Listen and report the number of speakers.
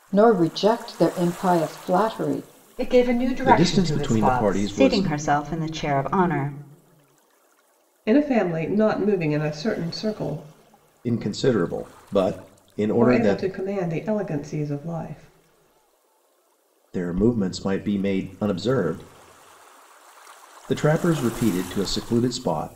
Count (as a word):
five